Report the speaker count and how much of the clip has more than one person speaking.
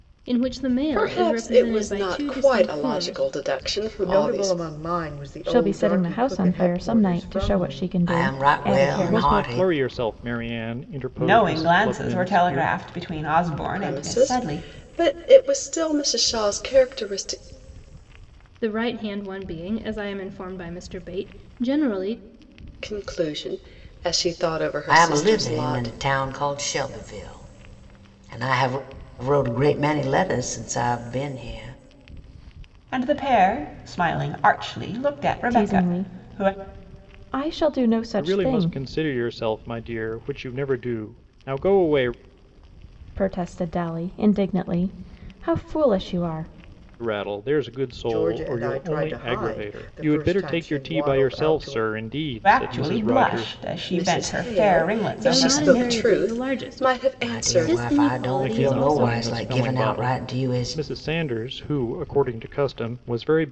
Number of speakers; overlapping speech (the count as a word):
seven, about 38%